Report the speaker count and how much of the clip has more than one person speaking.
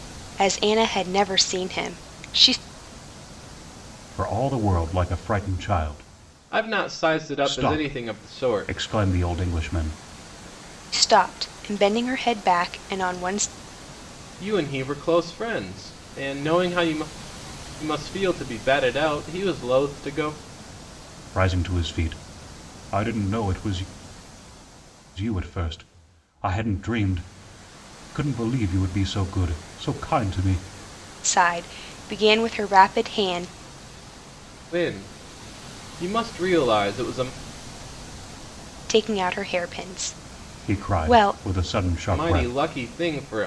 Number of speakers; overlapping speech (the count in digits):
3, about 6%